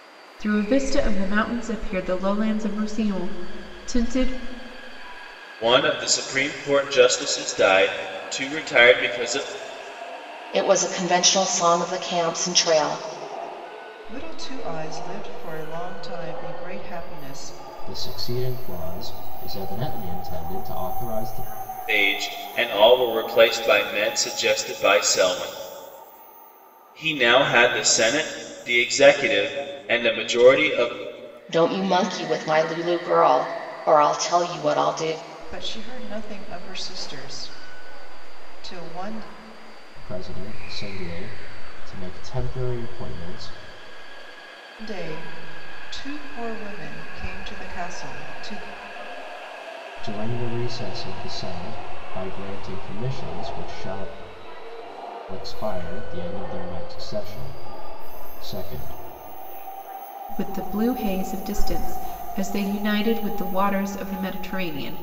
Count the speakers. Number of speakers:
5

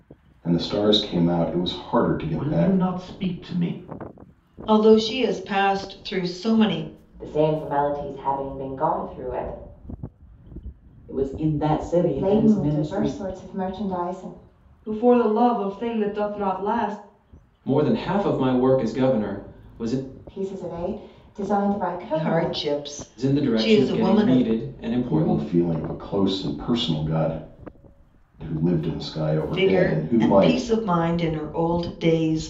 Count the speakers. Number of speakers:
8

